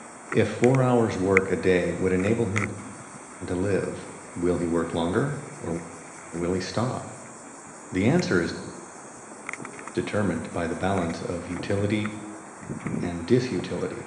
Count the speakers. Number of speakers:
one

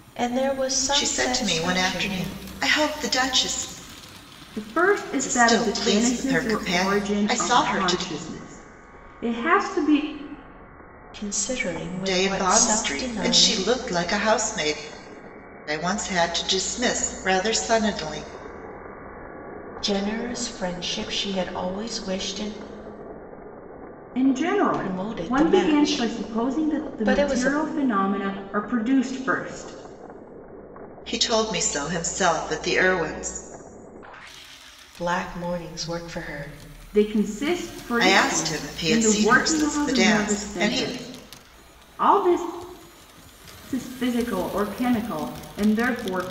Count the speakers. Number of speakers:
three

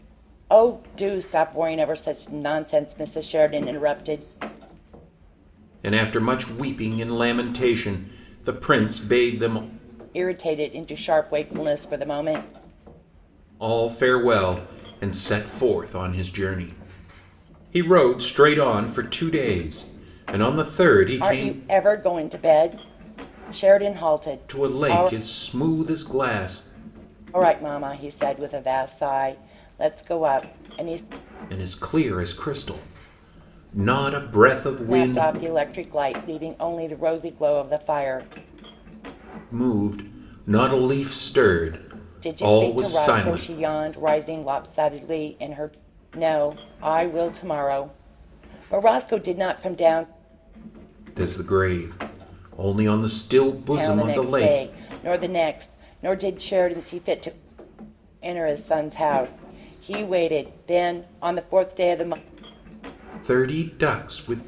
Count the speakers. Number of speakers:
two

